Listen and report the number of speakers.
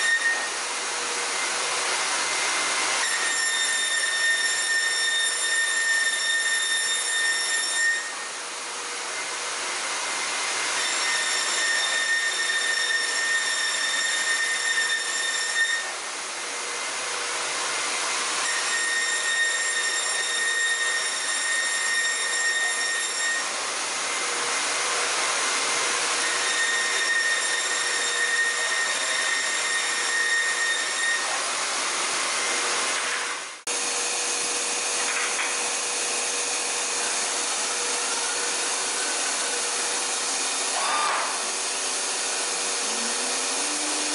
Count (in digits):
0